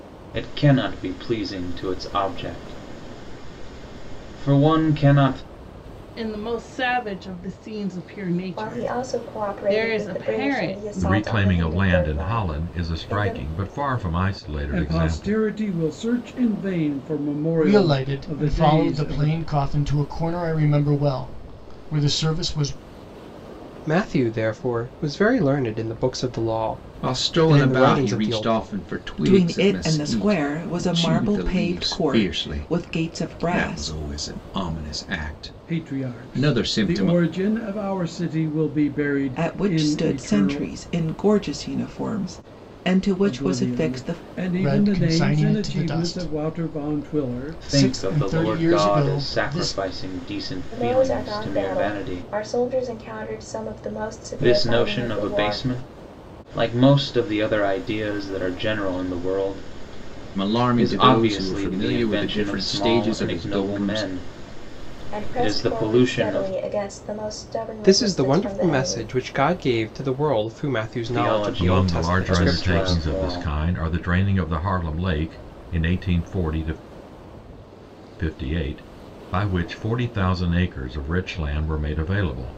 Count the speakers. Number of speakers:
nine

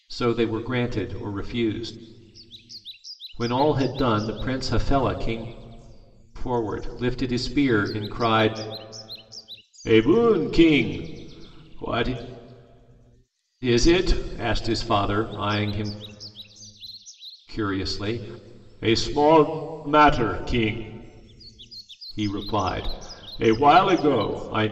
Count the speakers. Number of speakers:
one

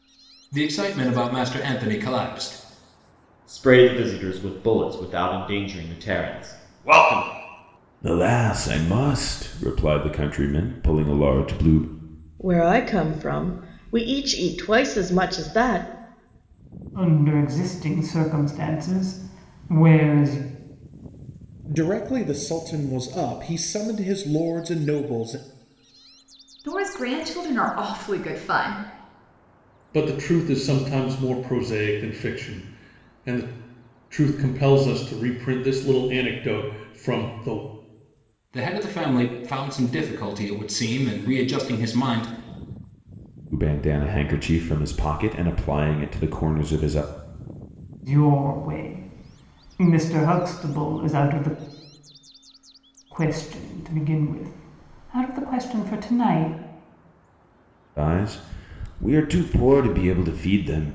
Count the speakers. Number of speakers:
eight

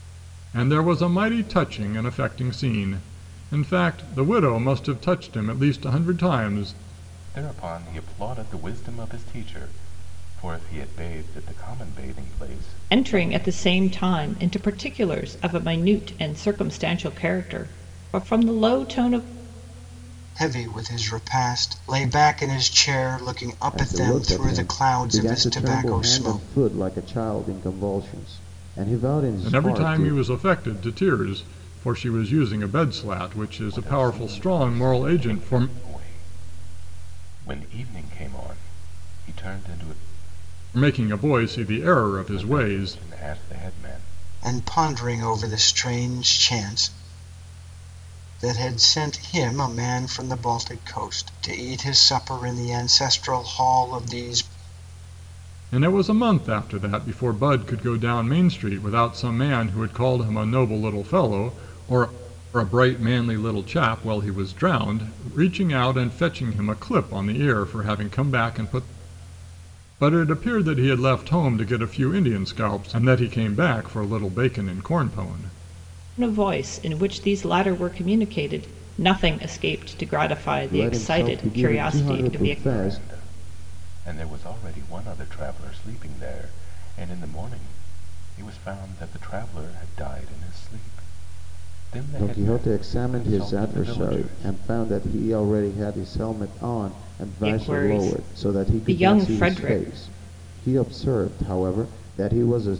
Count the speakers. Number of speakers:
five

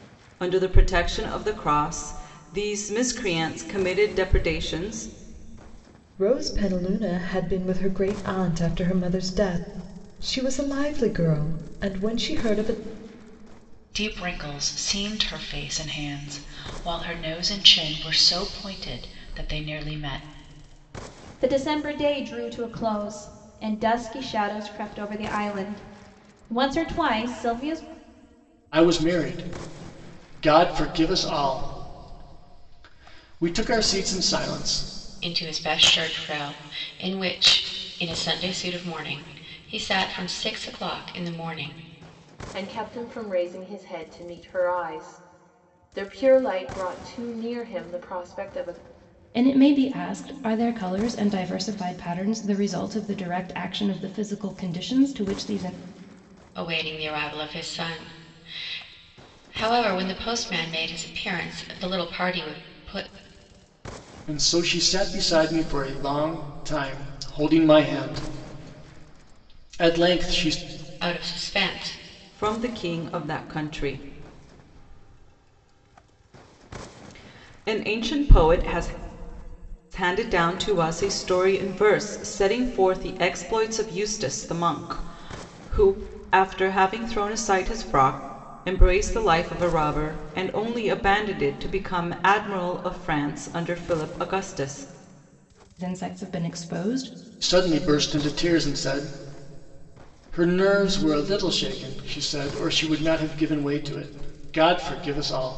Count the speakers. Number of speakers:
eight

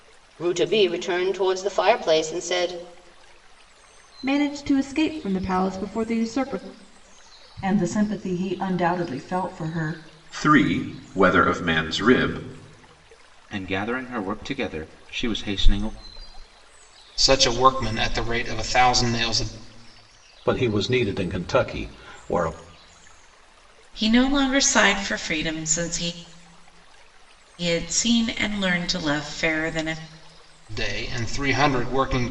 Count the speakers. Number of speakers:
eight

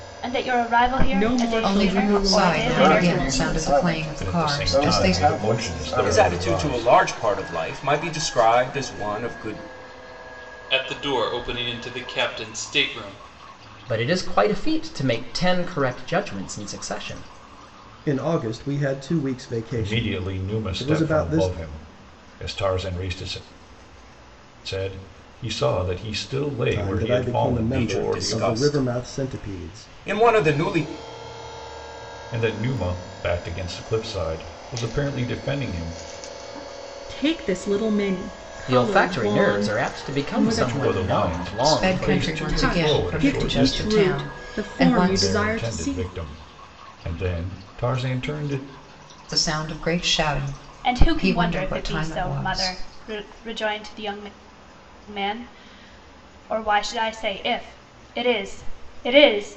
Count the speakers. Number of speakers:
nine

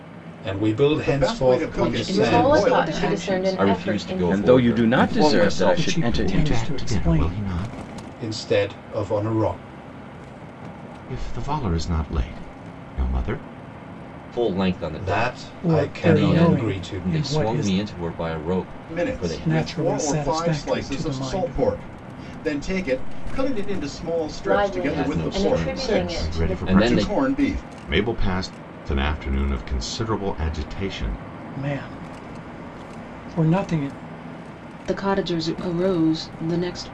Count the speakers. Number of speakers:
nine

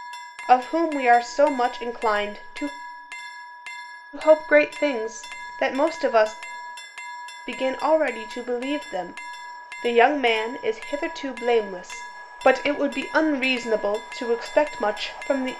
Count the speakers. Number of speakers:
one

